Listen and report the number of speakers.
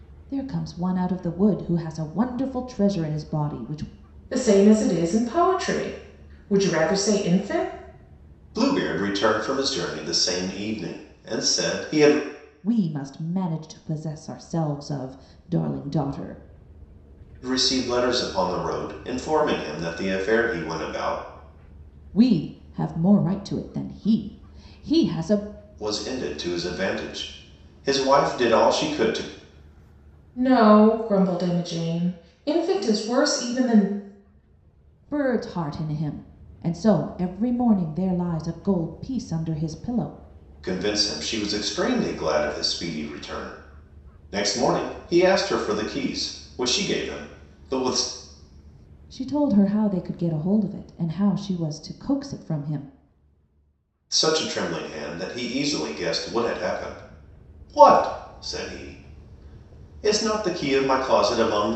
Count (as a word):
three